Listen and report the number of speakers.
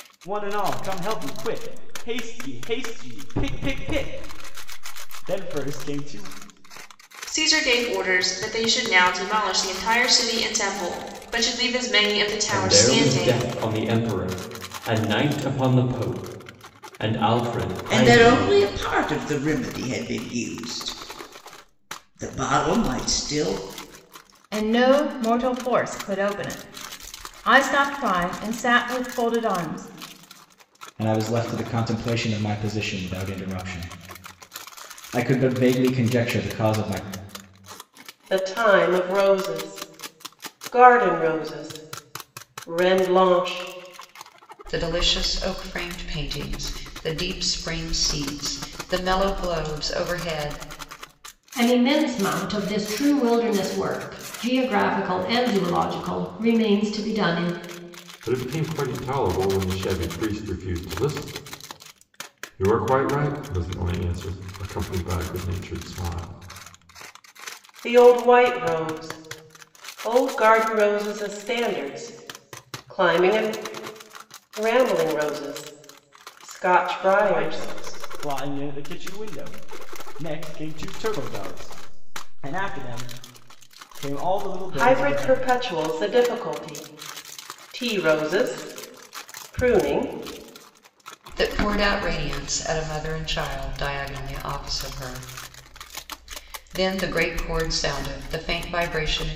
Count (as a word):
ten